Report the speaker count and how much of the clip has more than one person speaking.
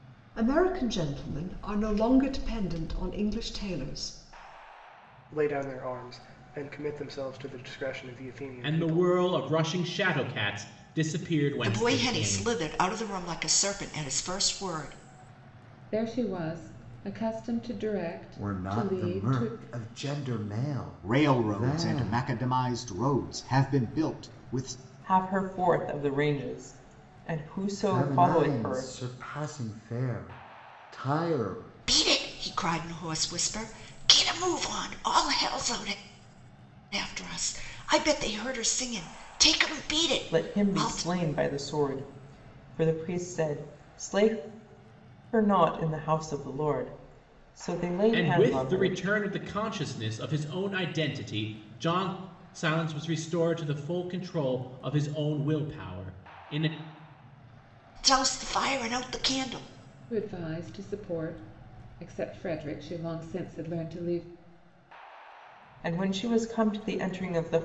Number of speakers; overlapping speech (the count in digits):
8, about 10%